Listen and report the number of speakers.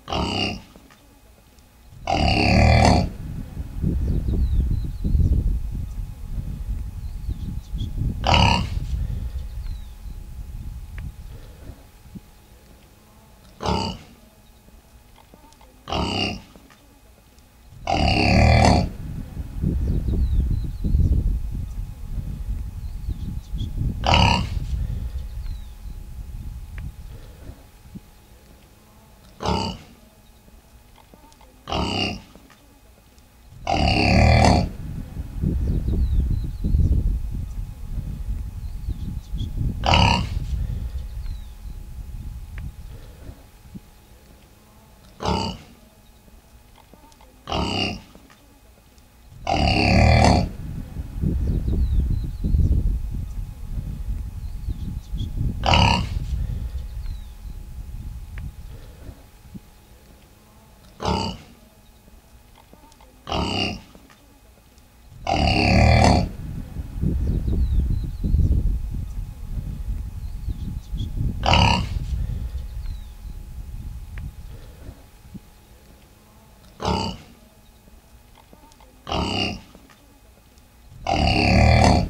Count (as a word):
zero